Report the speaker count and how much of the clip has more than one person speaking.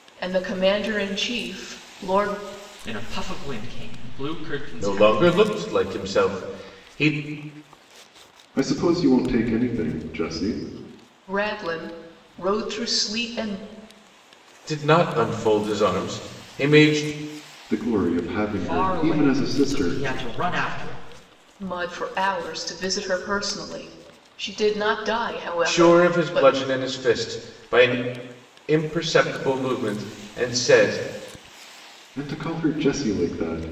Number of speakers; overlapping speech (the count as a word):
four, about 8%